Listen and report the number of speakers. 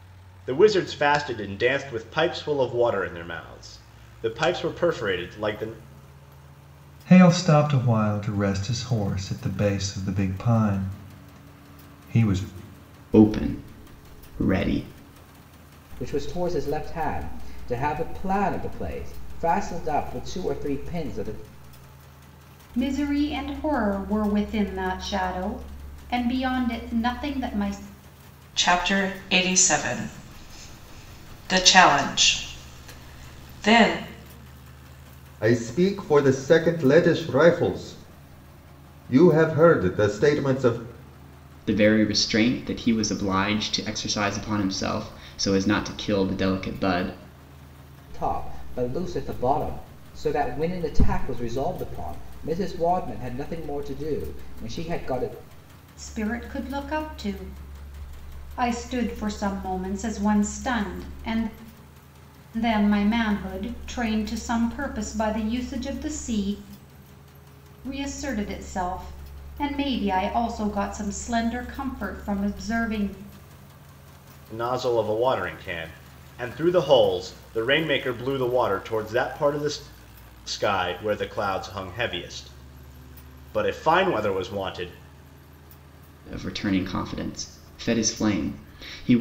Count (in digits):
7